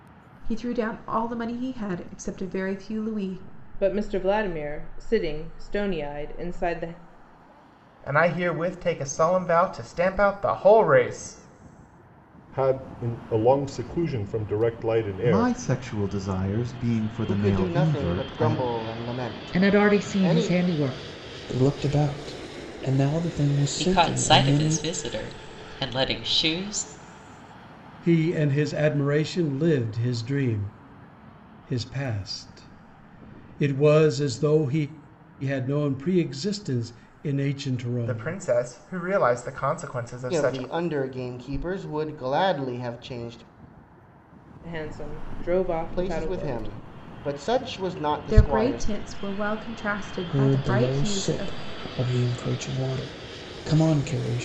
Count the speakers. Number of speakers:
10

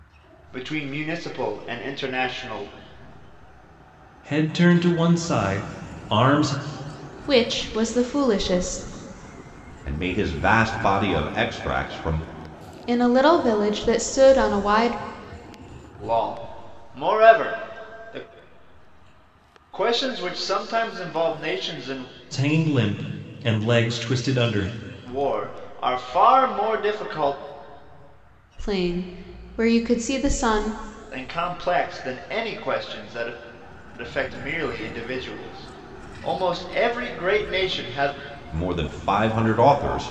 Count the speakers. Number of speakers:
4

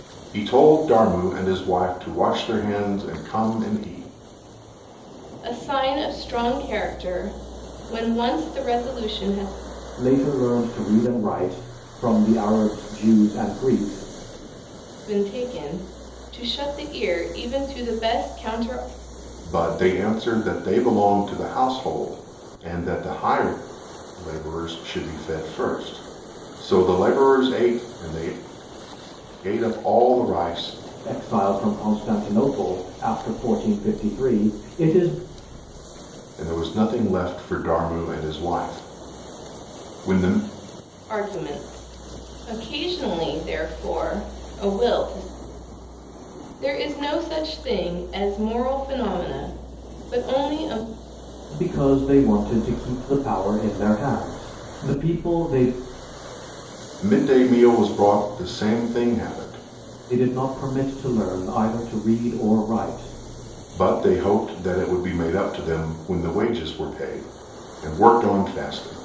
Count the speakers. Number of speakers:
3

